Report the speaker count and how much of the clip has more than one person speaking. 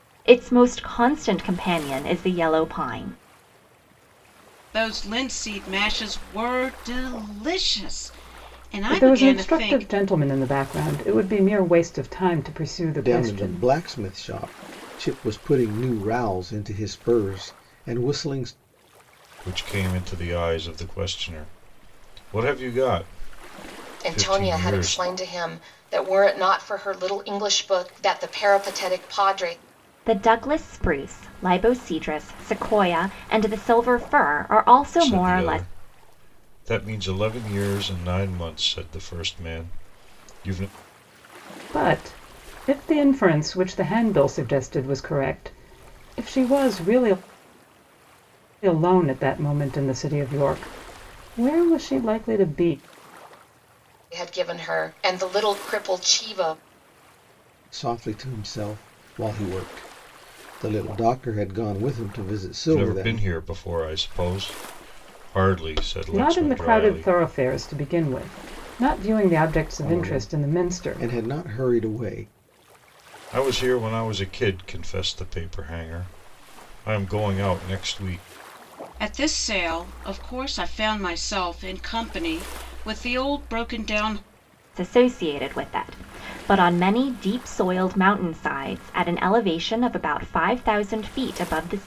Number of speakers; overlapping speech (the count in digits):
6, about 7%